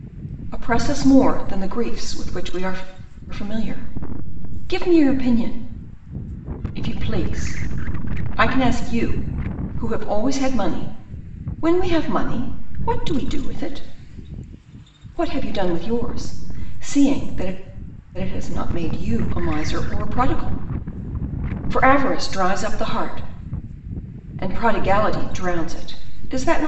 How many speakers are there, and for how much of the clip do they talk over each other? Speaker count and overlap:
one, no overlap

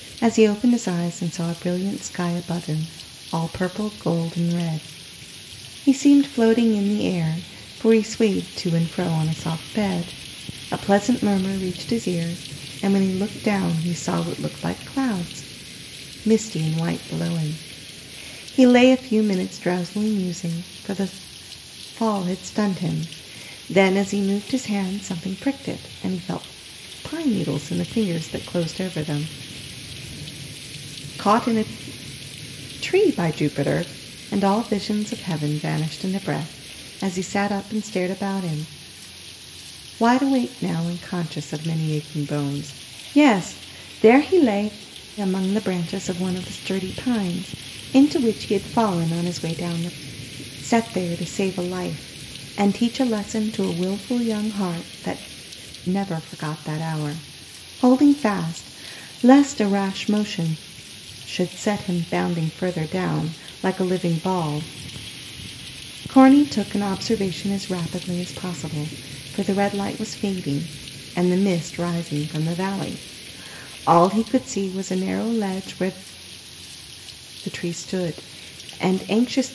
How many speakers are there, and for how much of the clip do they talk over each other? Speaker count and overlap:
one, no overlap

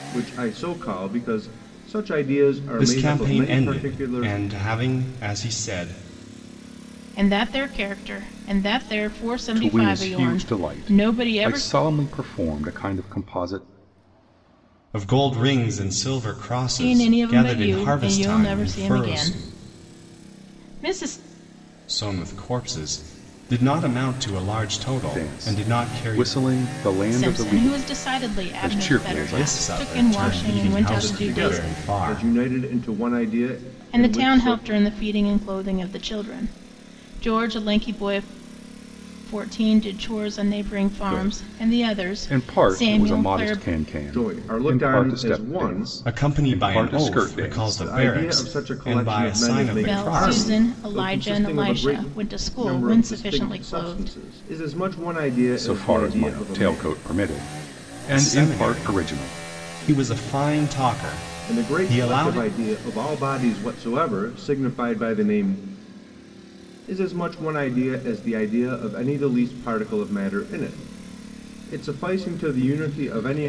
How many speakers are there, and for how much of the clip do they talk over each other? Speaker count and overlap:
four, about 40%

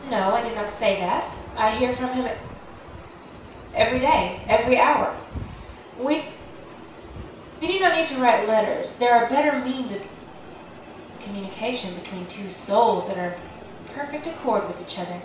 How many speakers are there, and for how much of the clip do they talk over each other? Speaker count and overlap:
one, no overlap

